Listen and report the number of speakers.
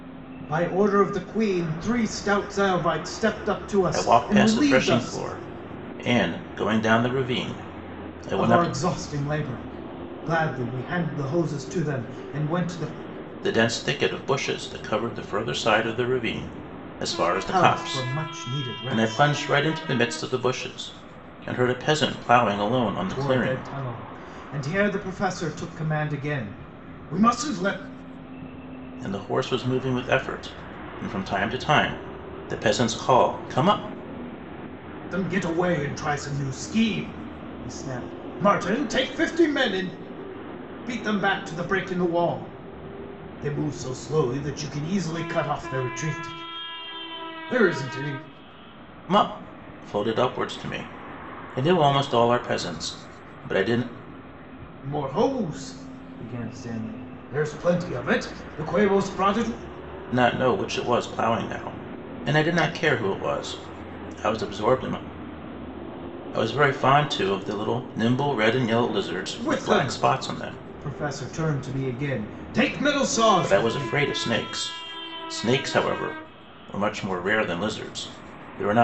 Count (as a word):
two